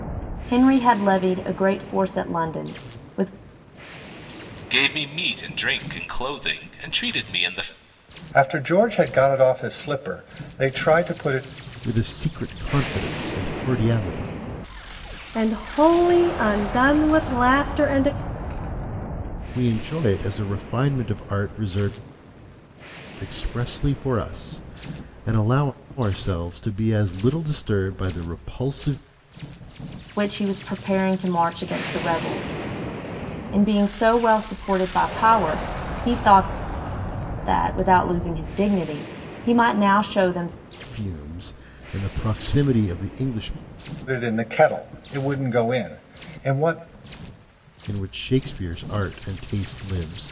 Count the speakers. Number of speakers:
5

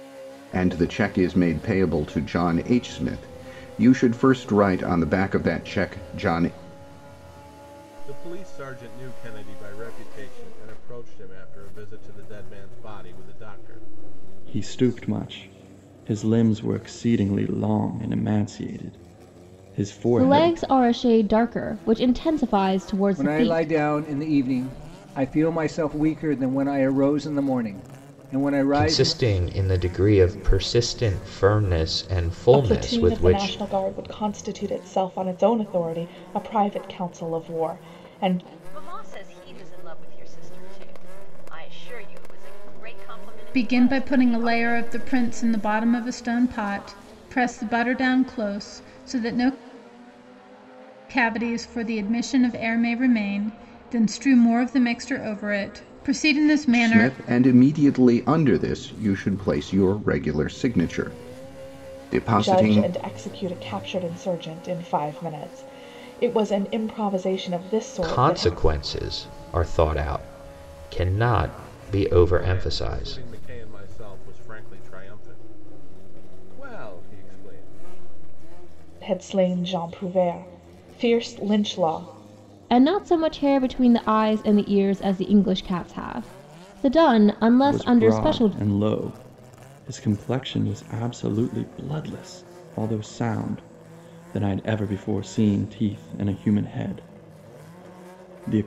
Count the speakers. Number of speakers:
9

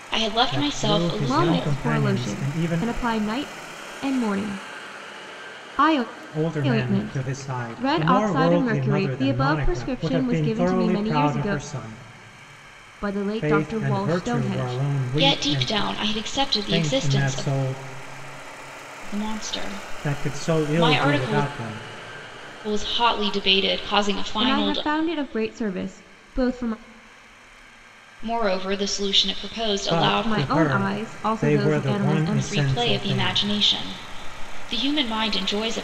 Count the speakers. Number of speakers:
3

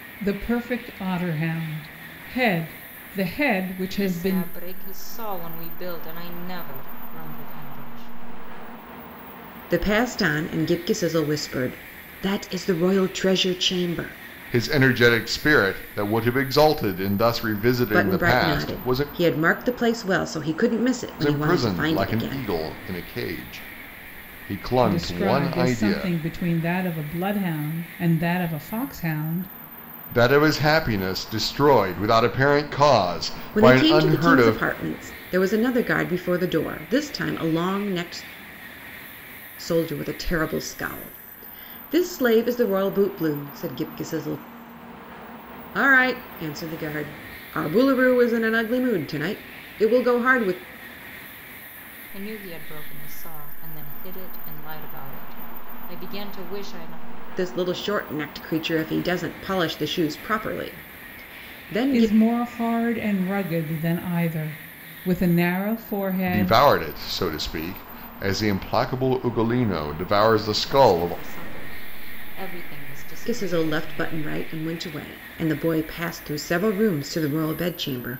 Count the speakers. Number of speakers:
4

